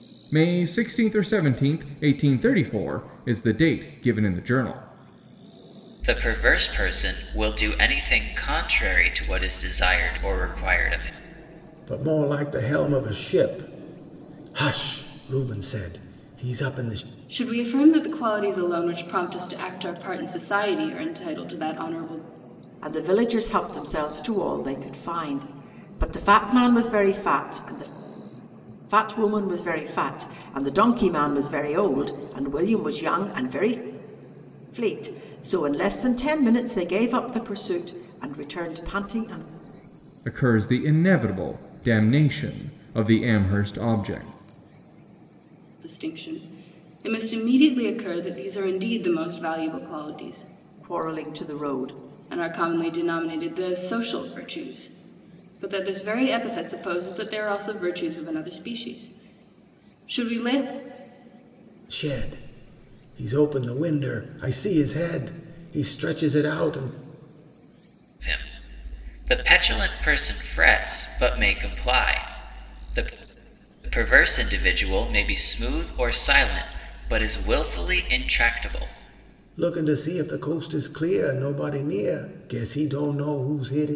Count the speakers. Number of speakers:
5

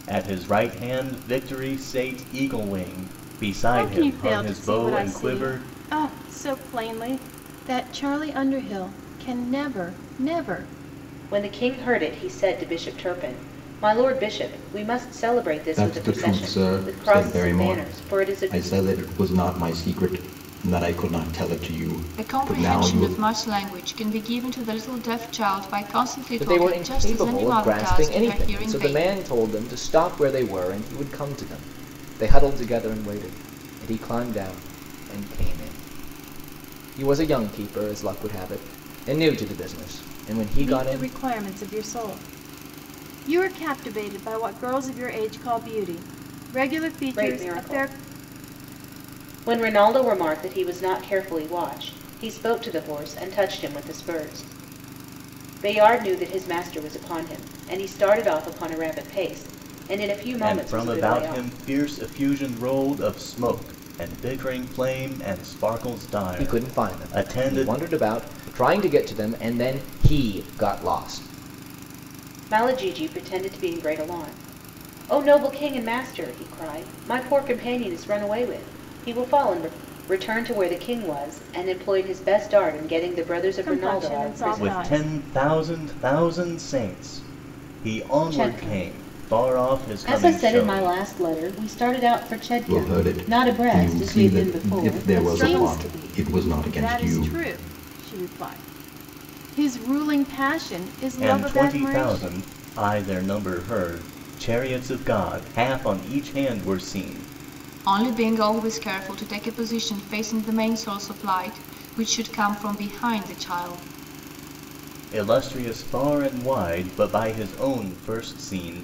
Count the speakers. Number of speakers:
6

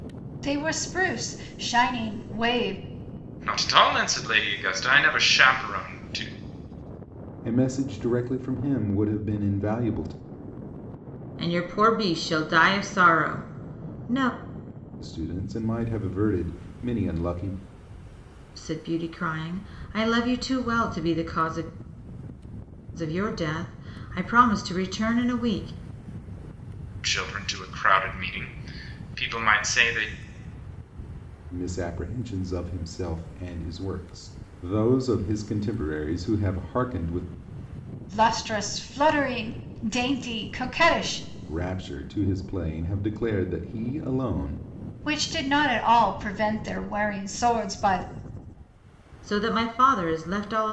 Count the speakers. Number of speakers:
4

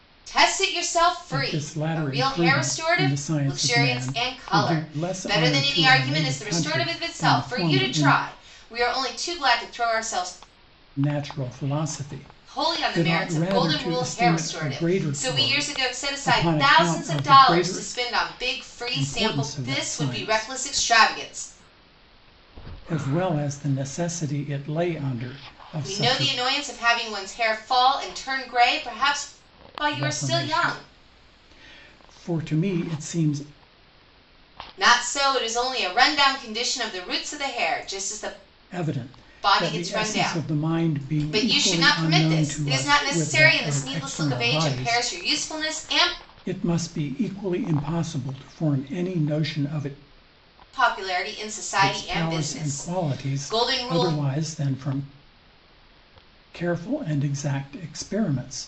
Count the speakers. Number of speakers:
2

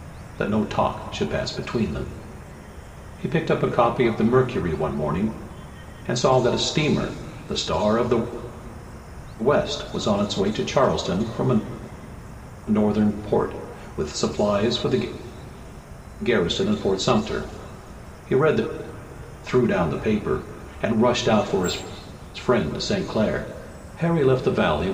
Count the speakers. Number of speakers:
1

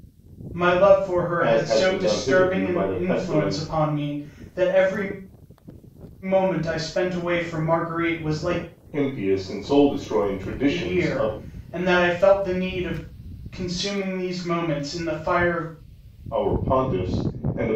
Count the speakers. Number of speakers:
2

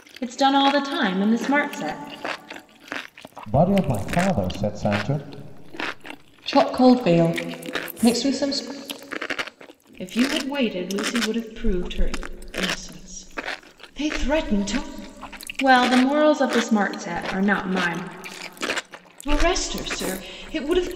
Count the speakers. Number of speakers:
4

